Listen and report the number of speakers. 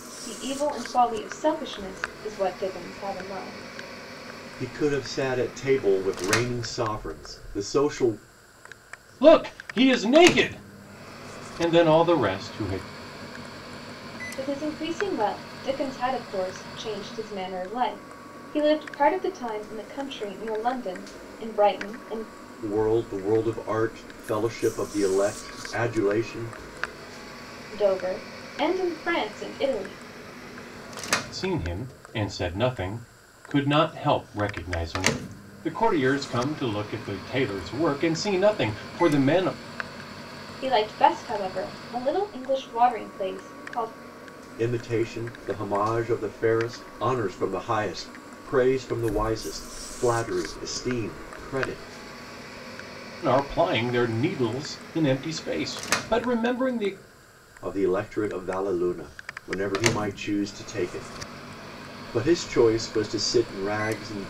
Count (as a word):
three